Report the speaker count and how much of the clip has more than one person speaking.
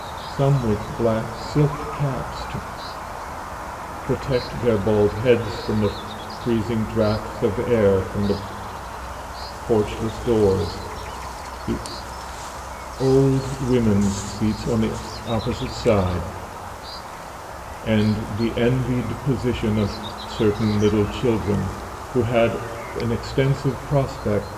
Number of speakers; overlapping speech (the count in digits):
1, no overlap